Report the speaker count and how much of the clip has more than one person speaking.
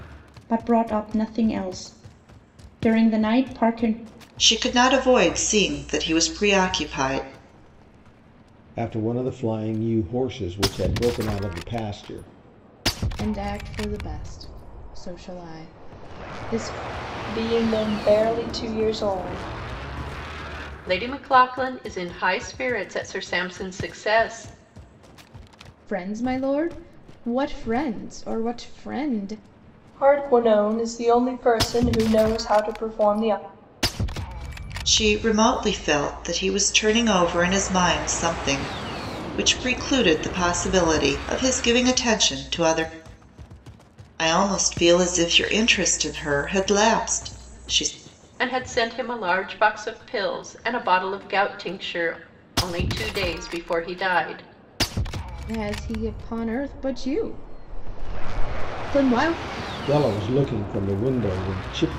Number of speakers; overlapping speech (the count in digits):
6, no overlap